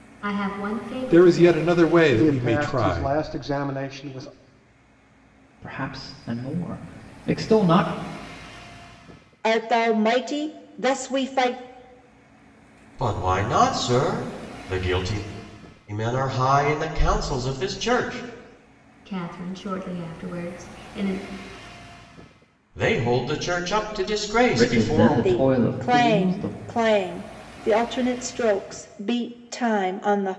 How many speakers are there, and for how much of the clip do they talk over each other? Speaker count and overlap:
six, about 14%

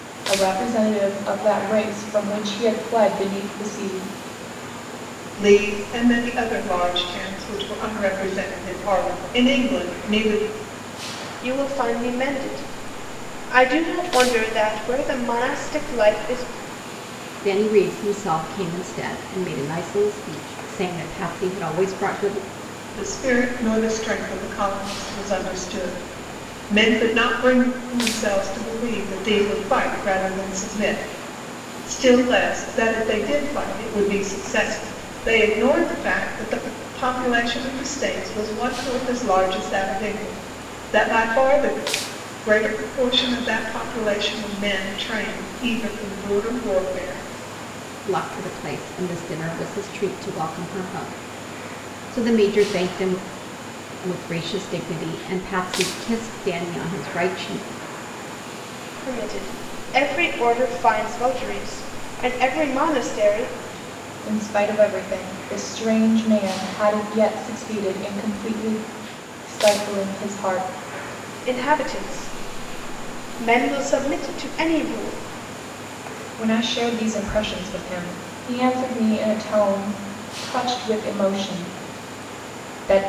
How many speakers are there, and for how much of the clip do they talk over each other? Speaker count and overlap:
four, no overlap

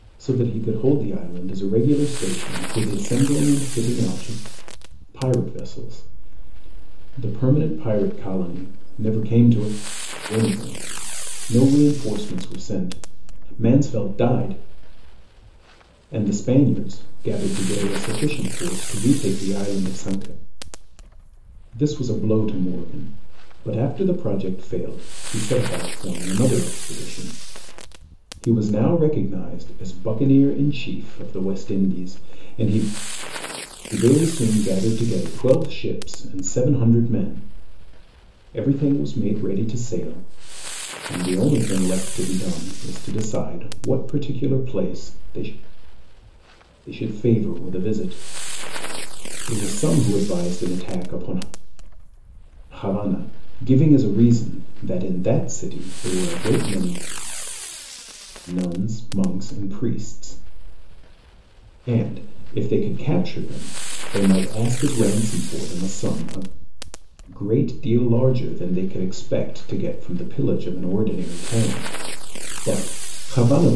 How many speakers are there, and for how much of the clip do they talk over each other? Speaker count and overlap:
one, no overlap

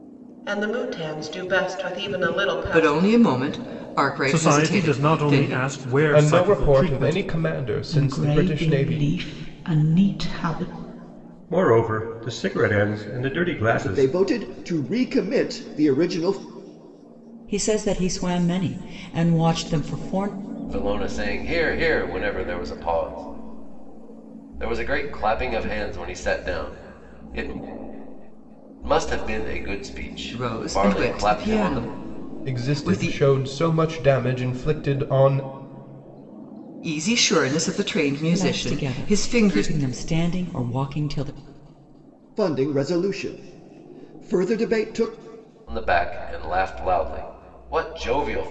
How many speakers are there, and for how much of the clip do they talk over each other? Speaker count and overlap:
nine, about 17%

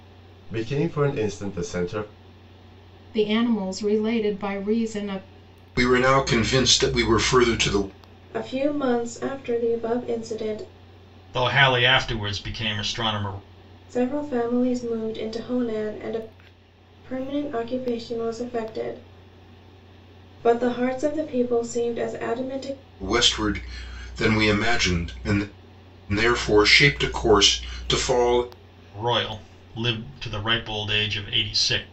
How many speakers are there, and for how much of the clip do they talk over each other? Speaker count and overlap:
five, no overlap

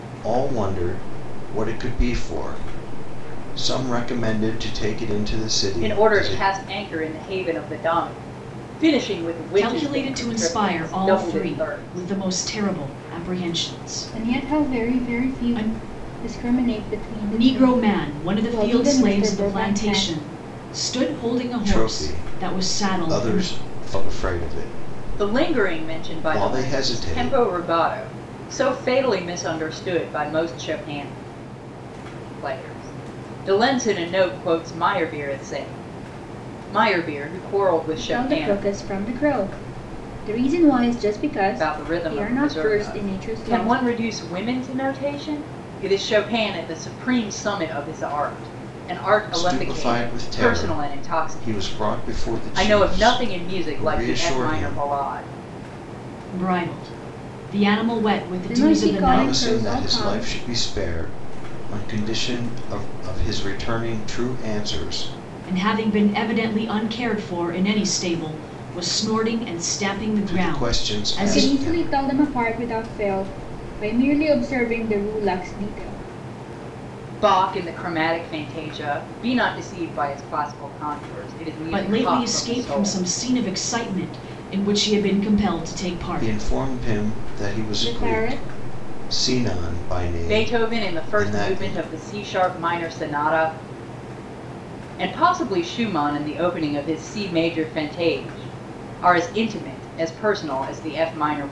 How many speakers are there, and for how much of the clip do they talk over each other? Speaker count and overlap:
four, about 29%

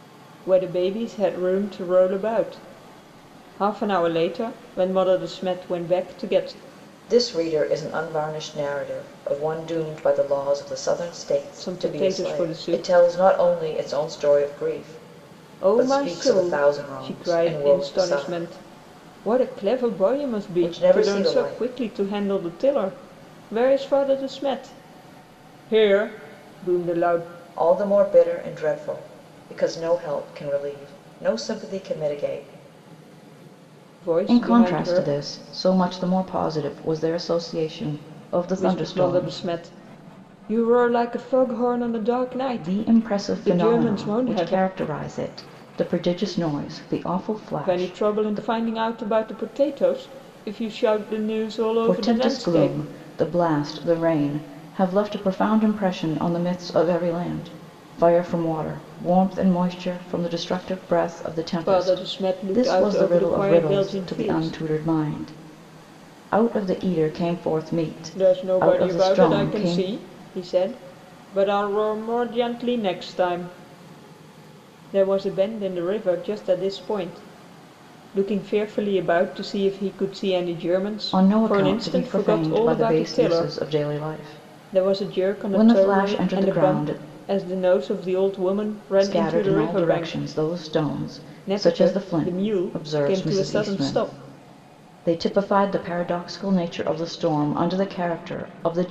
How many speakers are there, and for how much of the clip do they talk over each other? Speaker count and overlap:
two, about 25%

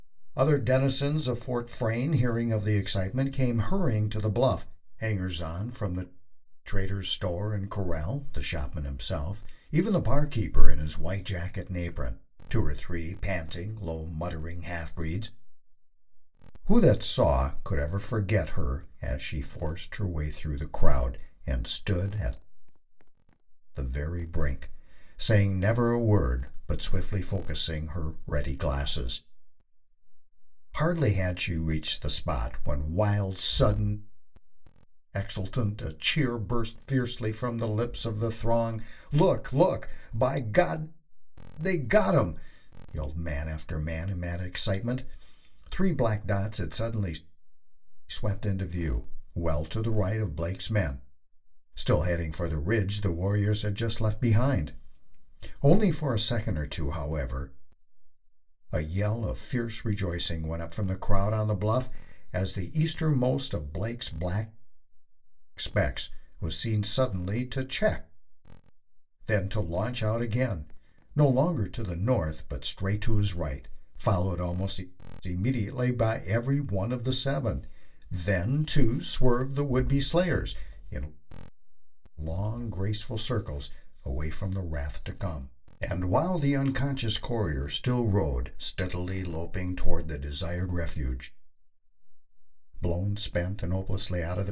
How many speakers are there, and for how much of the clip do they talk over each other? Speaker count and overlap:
one, no overlap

